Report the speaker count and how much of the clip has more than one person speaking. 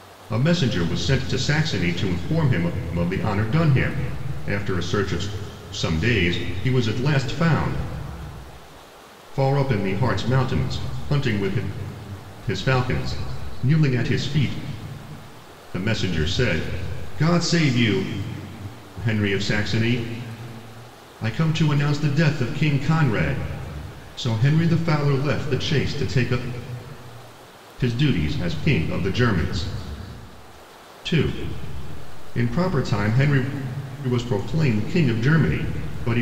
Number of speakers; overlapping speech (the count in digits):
1, no overlap